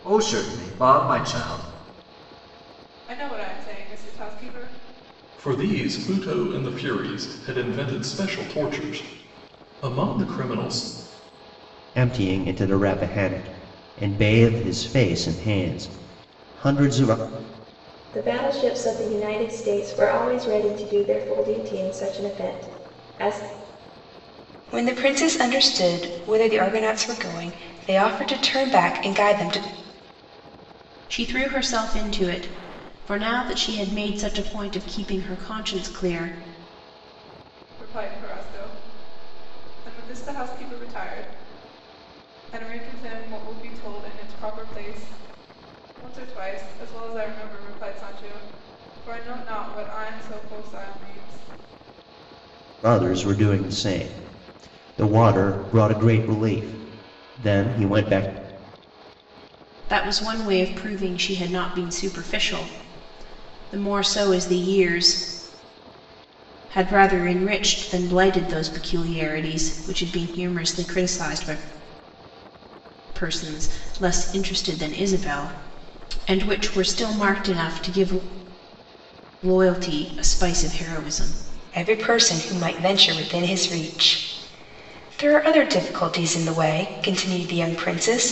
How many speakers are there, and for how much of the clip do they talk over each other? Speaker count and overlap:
7, no overlap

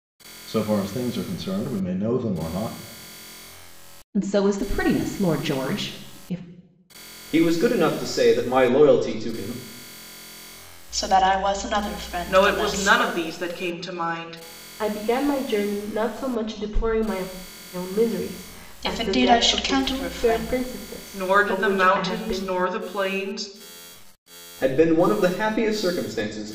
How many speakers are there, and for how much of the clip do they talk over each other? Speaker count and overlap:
6, about 15%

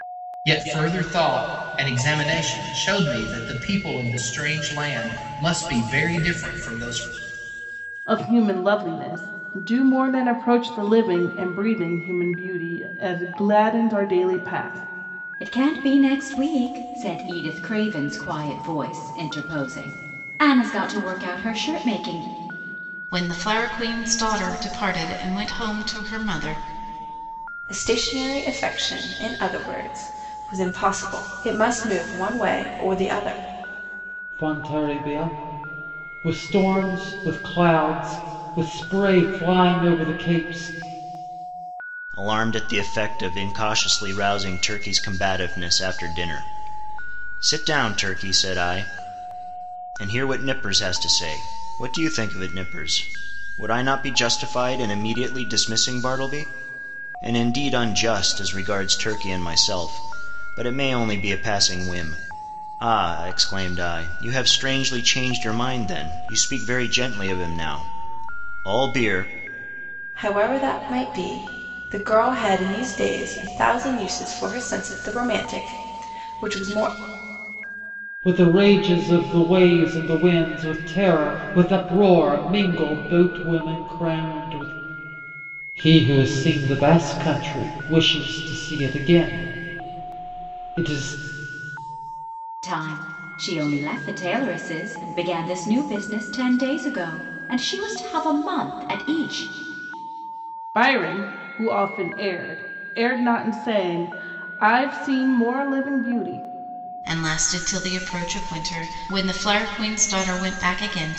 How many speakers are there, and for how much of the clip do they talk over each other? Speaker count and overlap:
7, no overlap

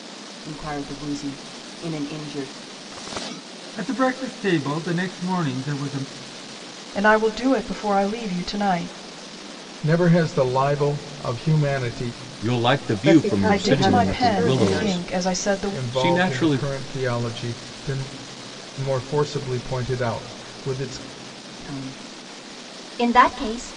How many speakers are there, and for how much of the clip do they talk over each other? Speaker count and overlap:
6, about 16%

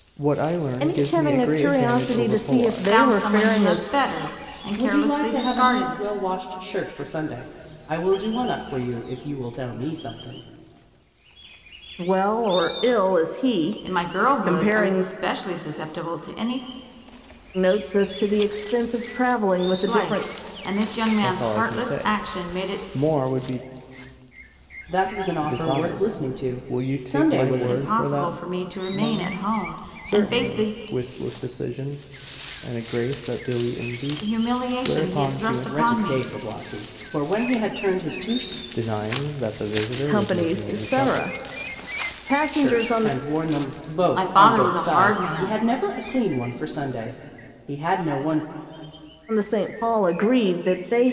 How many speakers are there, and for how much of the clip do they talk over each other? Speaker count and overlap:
4, about 36%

